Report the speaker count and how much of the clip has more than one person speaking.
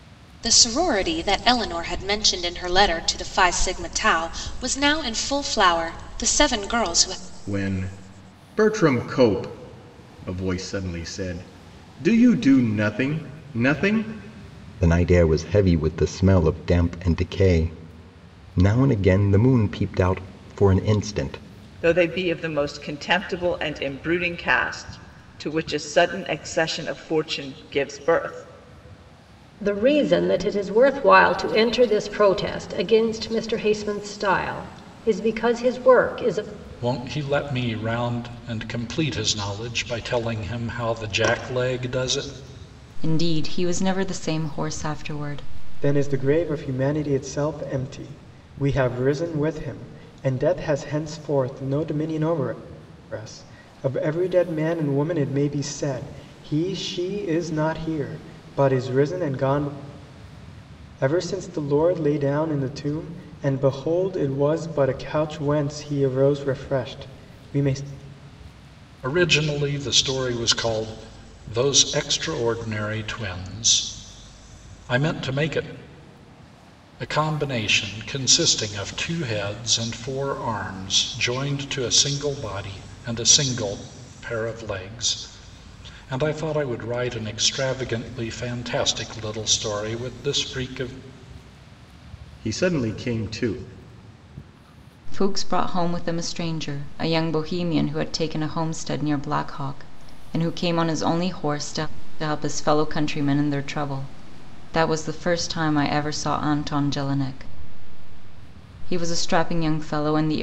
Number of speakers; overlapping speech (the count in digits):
8, no overlap